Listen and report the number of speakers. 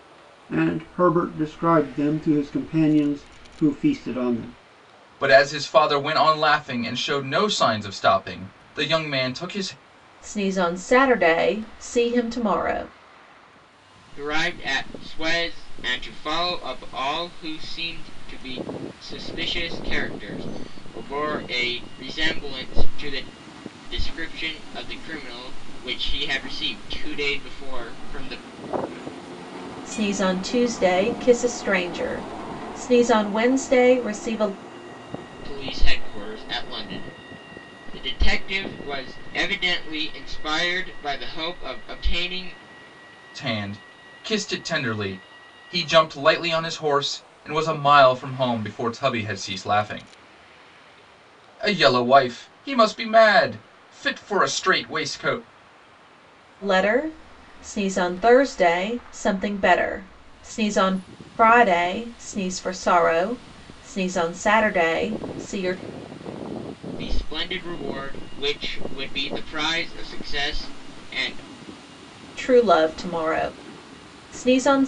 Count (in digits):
4